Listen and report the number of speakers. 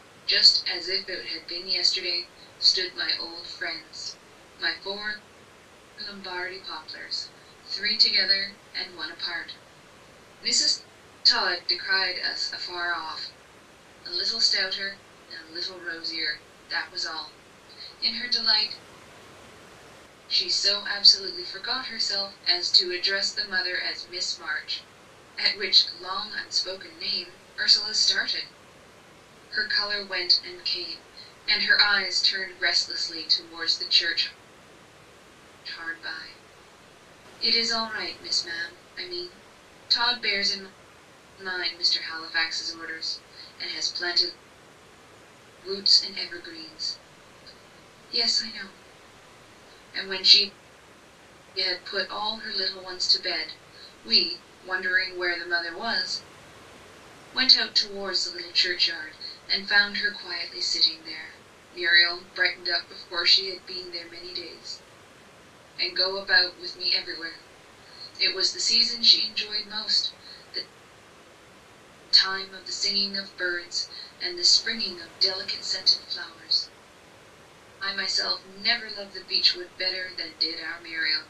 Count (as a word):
one